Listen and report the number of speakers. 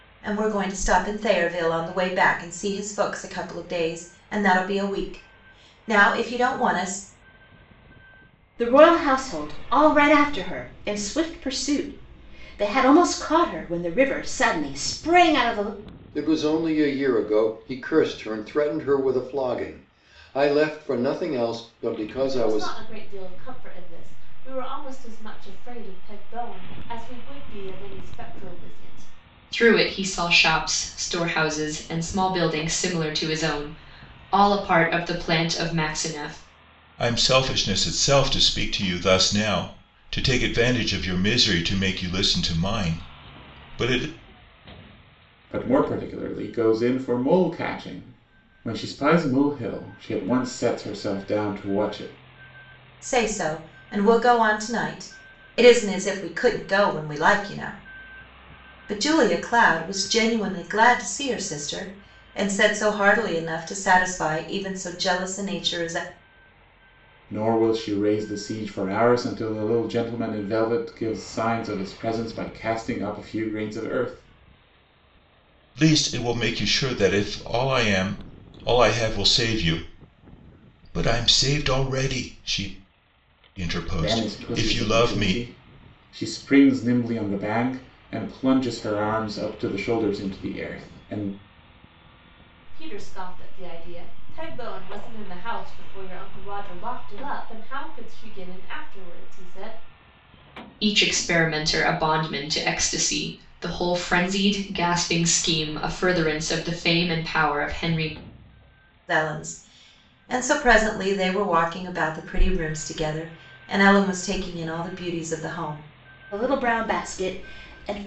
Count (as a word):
seven